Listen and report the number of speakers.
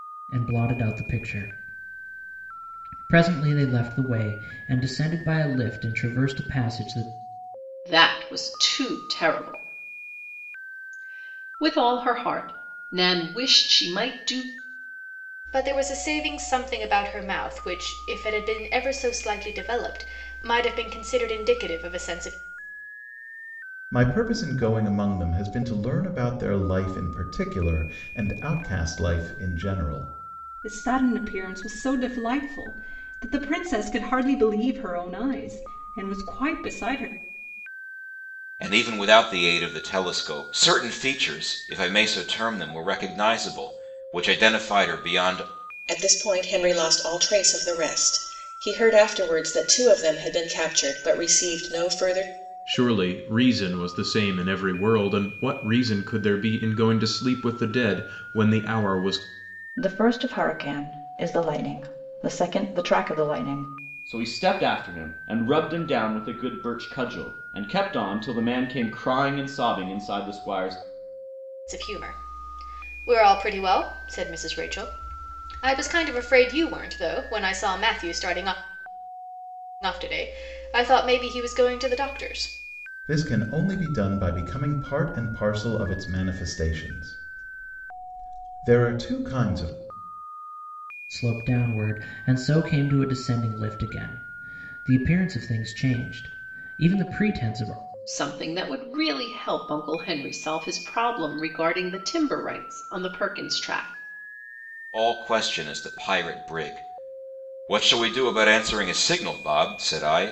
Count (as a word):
ten